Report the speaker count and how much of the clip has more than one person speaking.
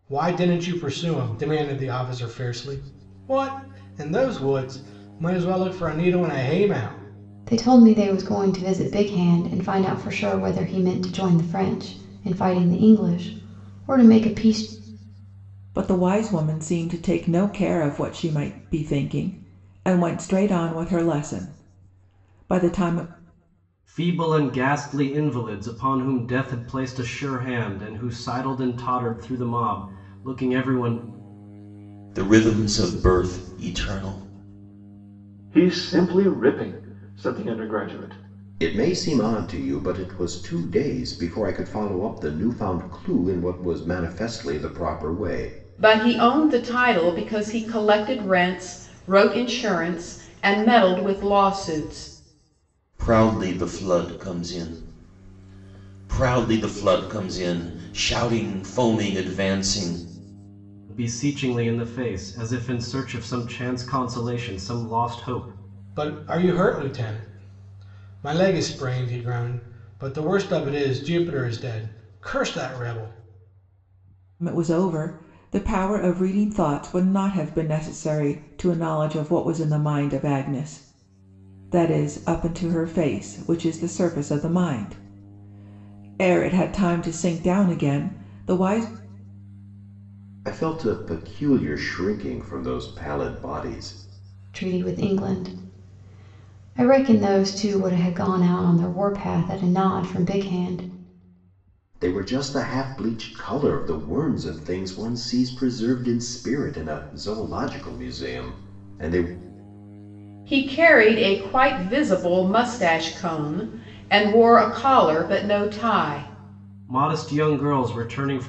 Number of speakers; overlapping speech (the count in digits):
8, no overlap